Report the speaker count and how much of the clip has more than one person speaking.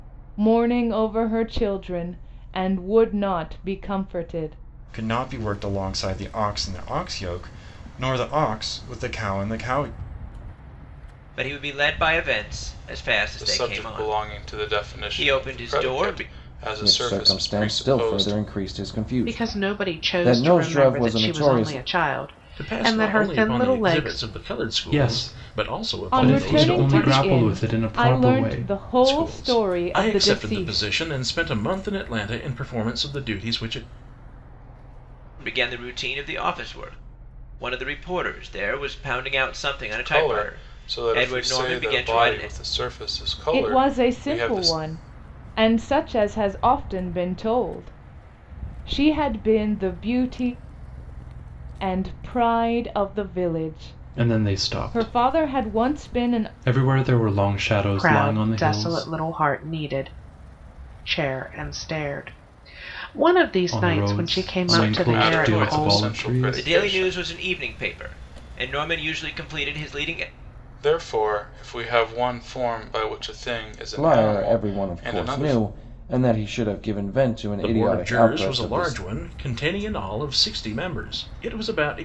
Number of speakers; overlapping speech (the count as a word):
eight, about 35%